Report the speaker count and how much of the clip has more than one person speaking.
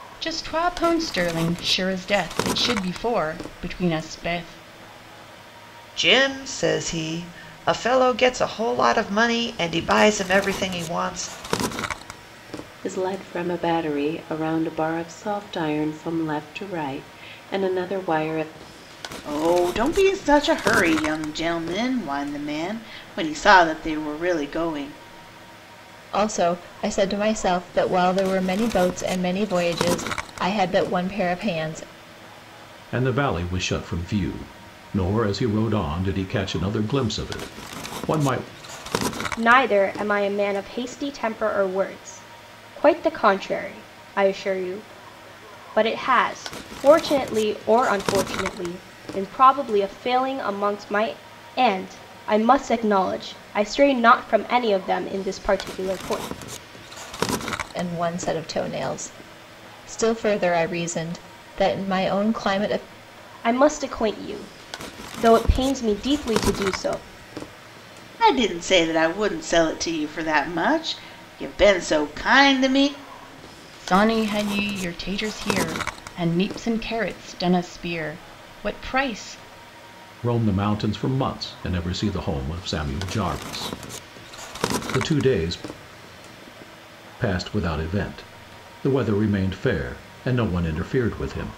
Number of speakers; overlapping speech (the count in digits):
7, no overlap